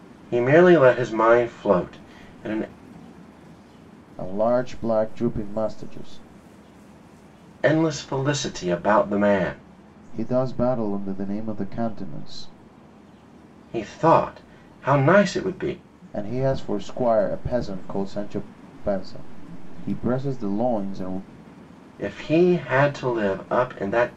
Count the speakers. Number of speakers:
2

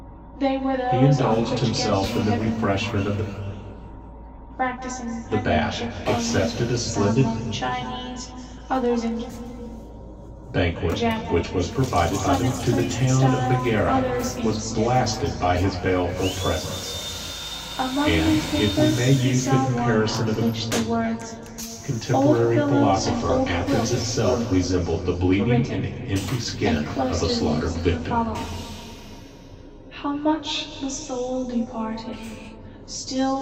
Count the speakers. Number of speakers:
2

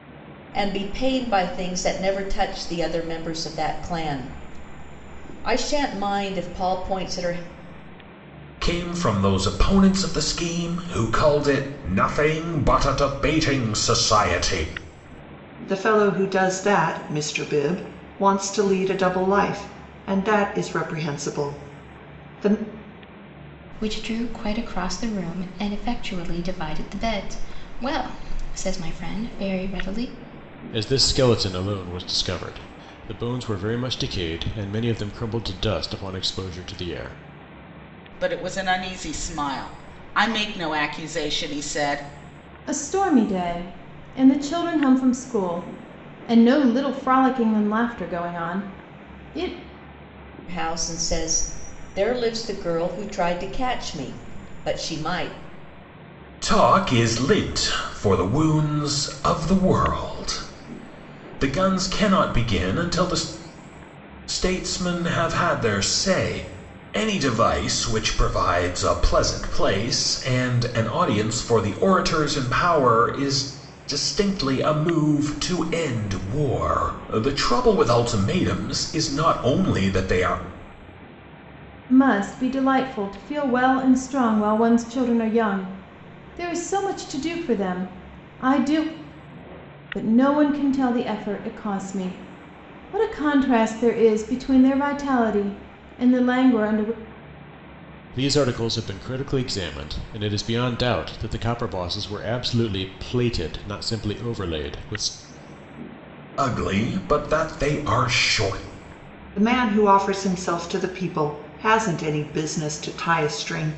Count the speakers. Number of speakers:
7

